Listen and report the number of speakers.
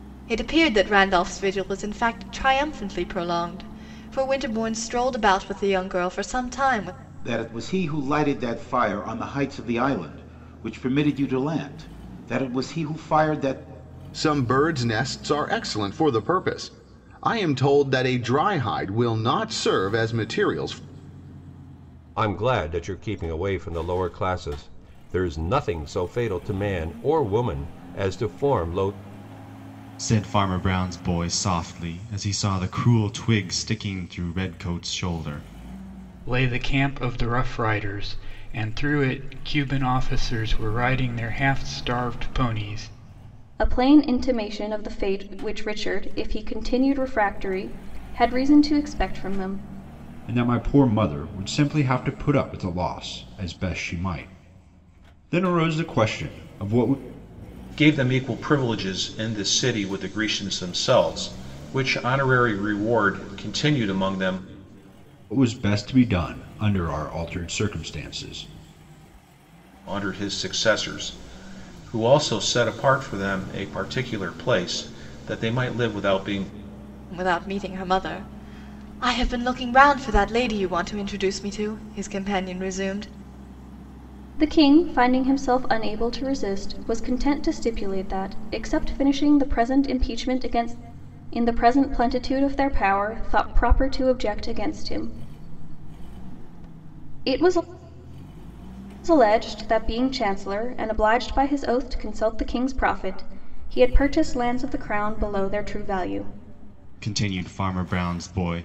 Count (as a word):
nine